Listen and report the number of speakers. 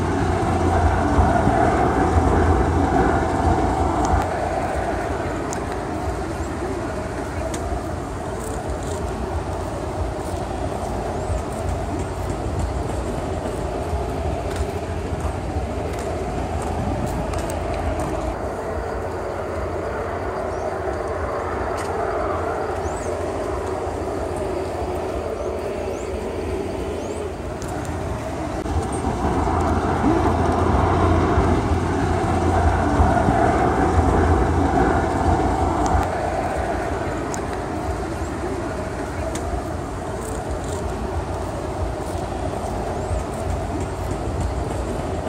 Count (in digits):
0